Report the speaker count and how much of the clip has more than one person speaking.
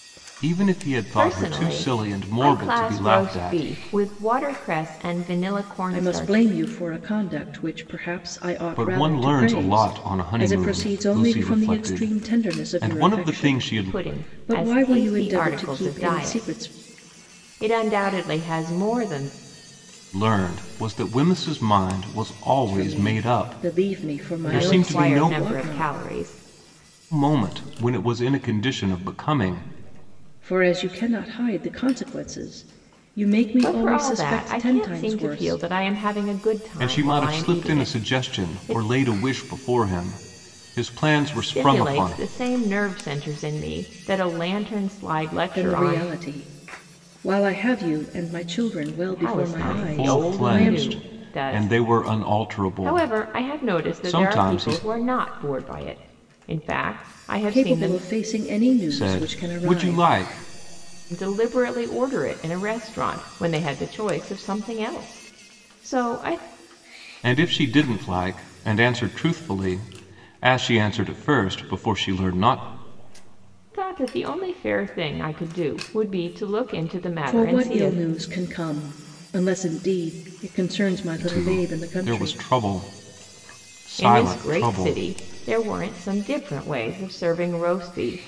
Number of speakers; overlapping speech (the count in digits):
3, about 34%